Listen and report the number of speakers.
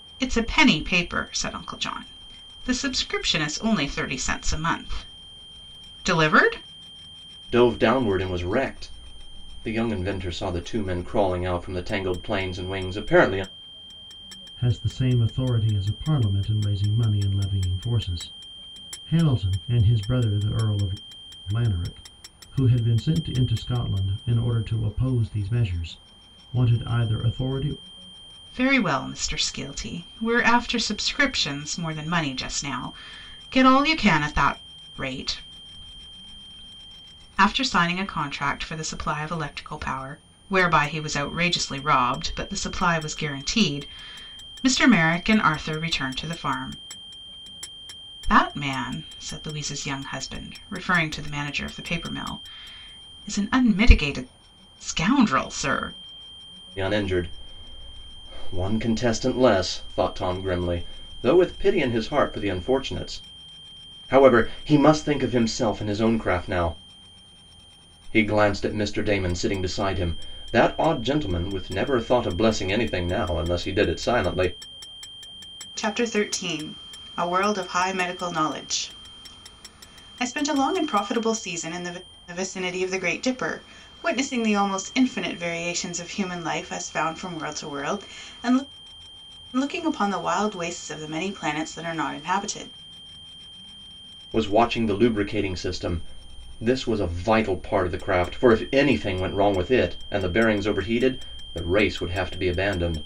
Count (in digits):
3